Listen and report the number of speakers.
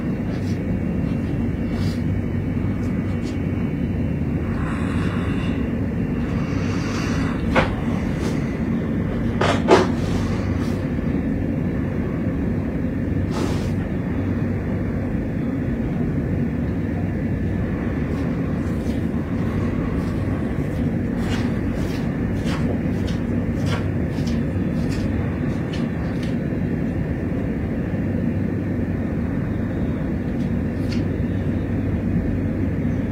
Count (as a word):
zero